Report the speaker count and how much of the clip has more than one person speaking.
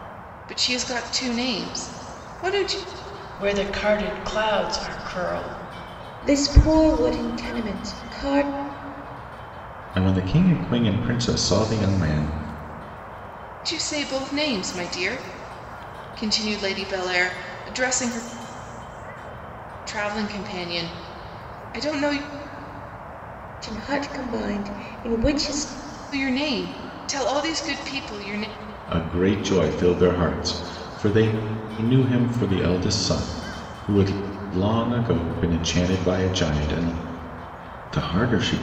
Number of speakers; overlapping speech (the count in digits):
4, no overlap